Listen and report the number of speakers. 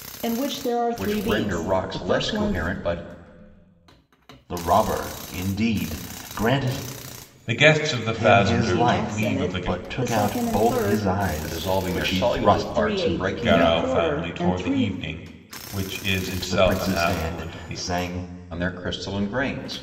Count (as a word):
four